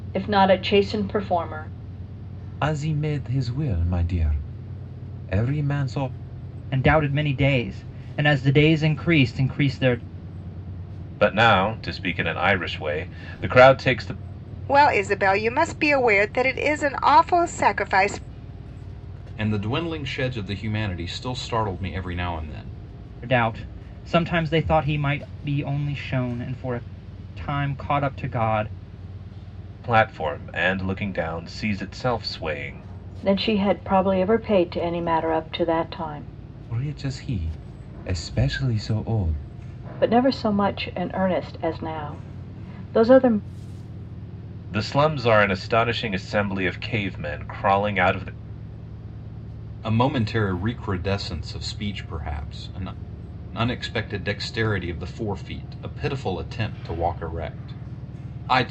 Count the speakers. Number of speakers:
6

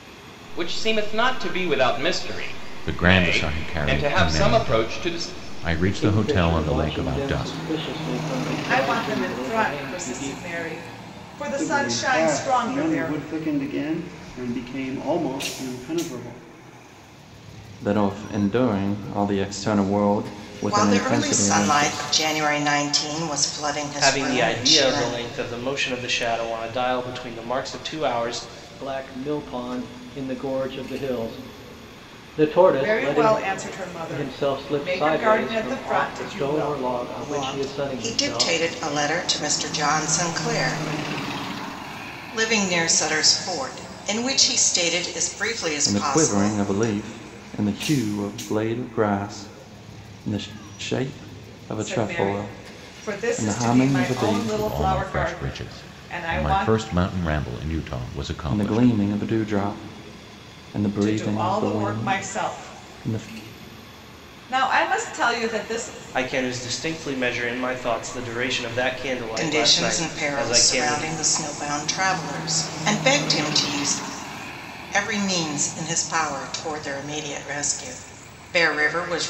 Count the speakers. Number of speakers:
8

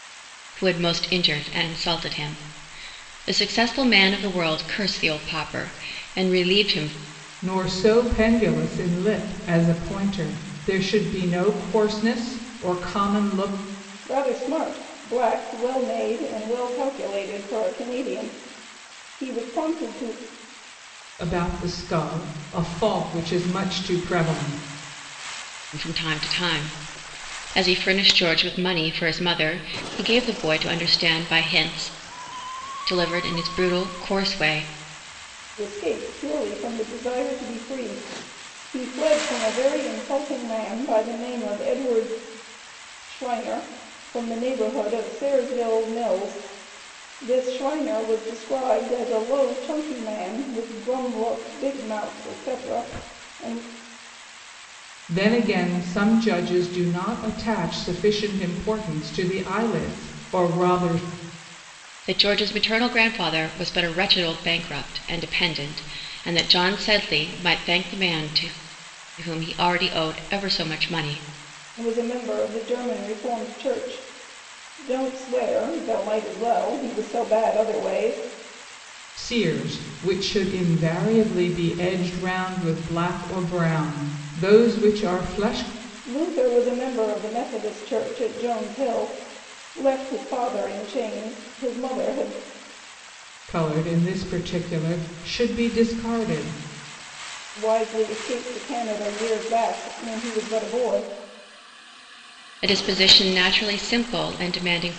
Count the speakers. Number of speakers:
3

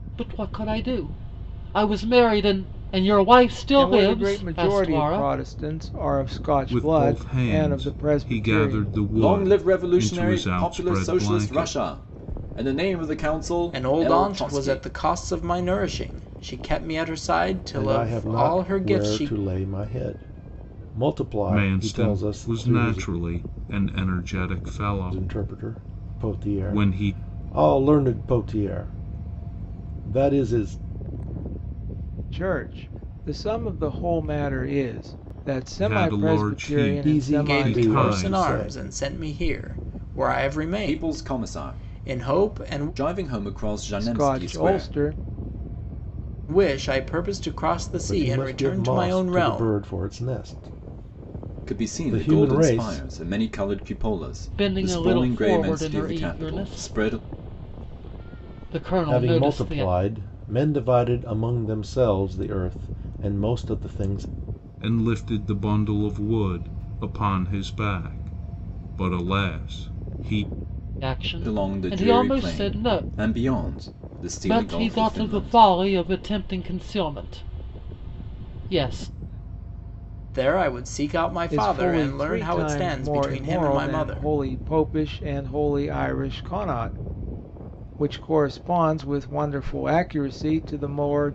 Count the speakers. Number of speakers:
6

